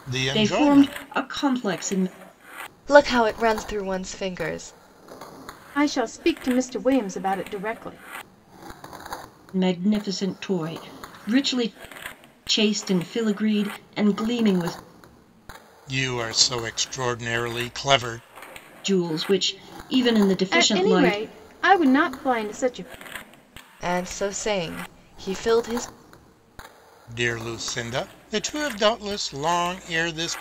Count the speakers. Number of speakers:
4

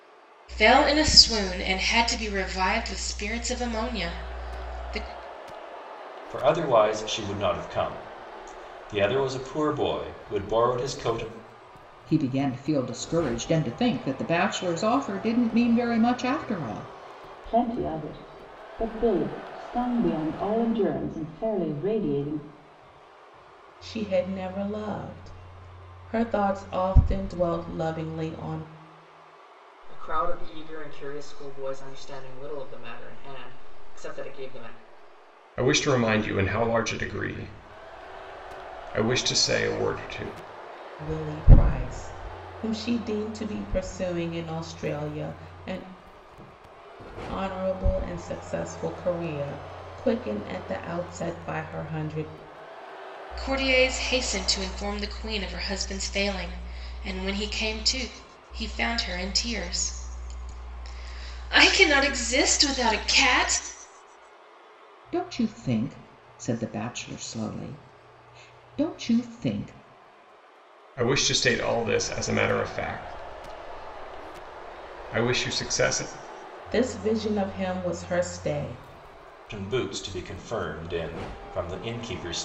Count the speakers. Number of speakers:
7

